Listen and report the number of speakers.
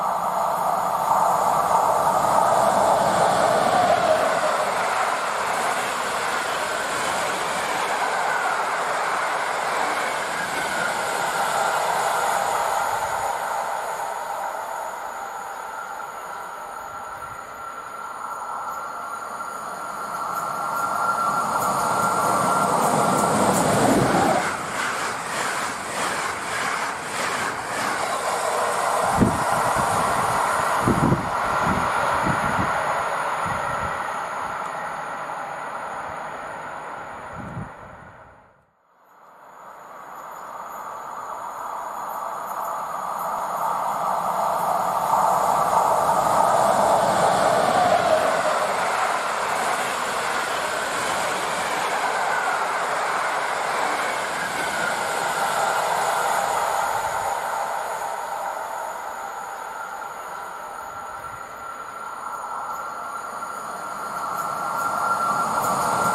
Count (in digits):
0